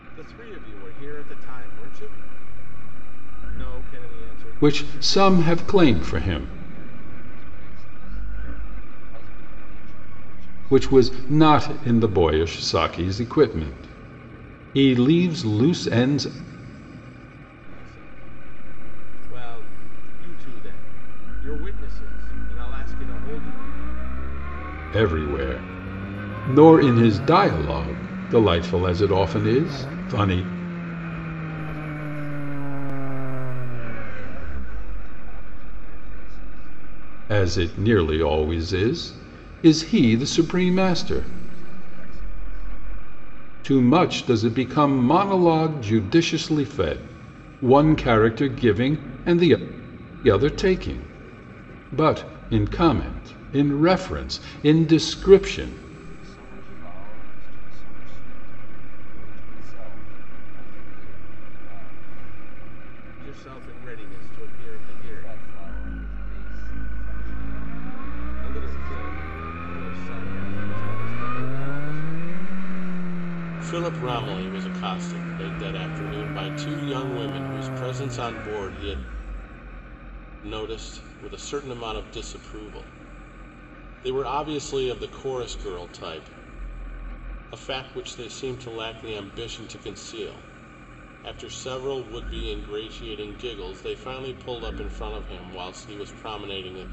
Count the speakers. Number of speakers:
3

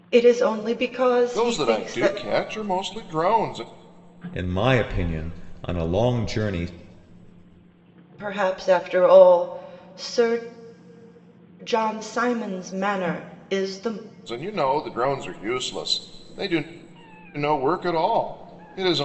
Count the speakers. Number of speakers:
3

